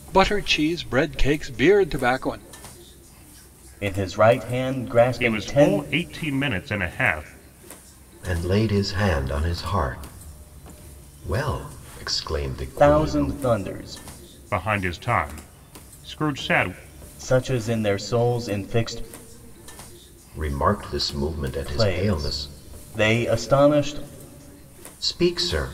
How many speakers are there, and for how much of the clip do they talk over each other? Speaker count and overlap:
four, about 9%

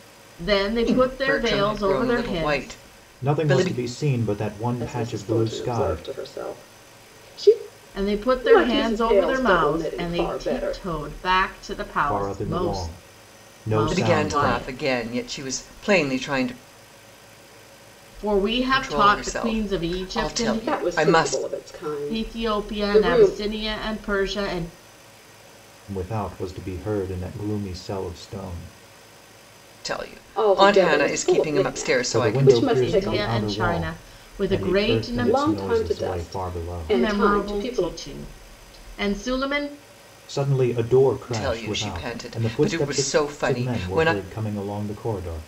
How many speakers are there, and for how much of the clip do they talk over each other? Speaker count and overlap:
four, about 50%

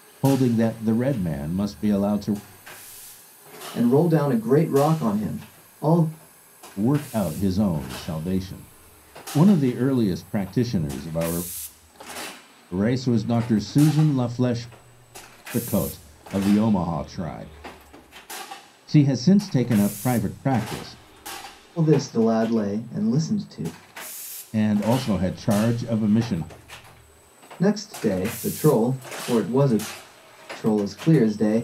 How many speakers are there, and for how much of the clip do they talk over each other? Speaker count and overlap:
two, no overlap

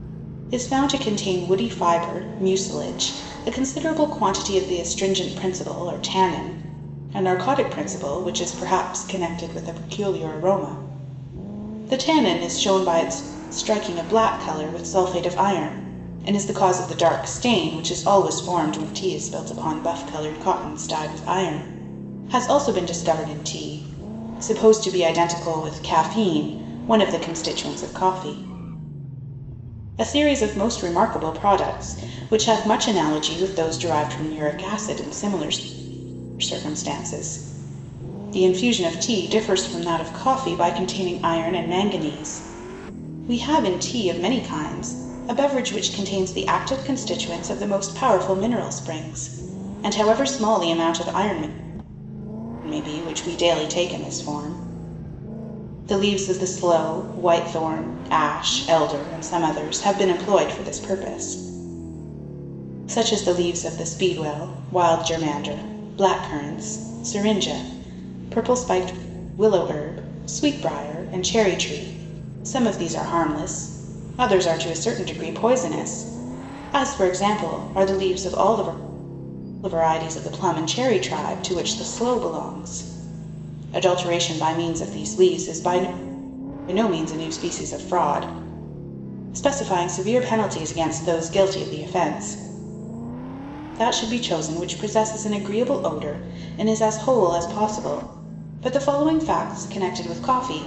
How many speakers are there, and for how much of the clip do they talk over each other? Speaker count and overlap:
one, no overlap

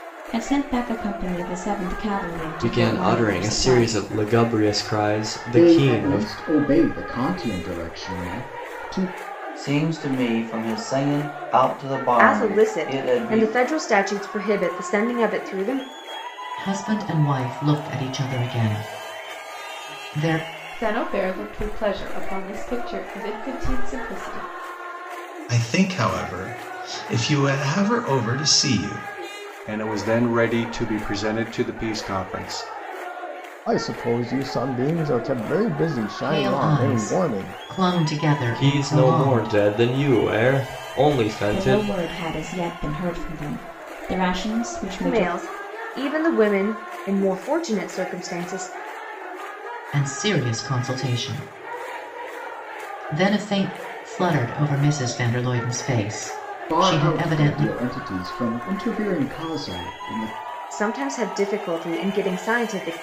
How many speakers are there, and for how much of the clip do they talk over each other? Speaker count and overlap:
ten, about 13%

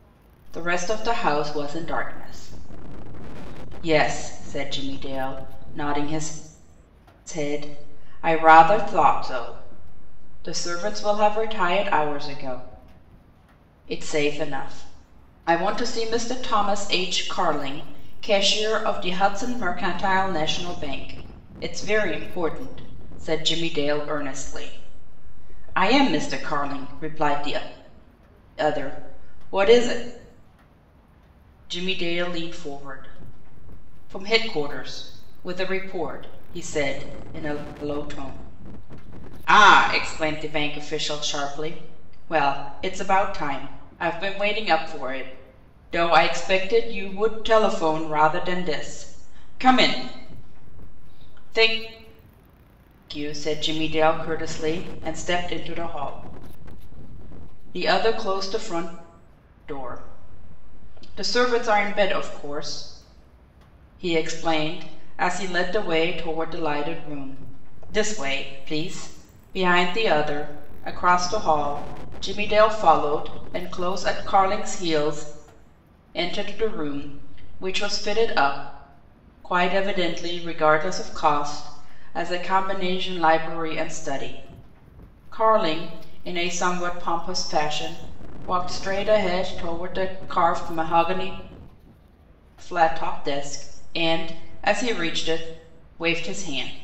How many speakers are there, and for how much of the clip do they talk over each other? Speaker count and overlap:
one, no overlap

